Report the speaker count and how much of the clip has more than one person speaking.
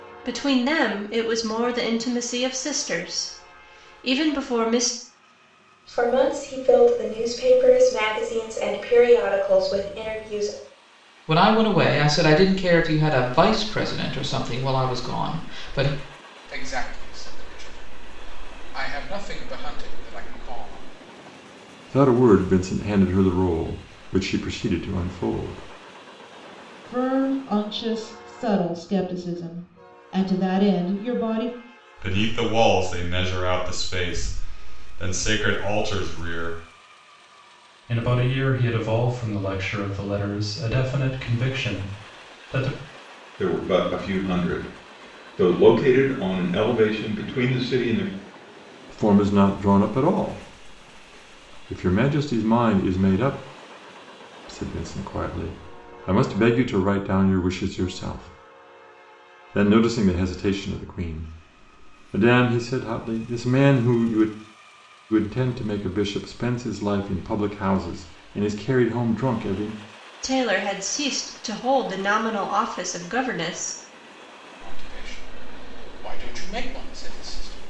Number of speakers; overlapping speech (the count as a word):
nine, no overlap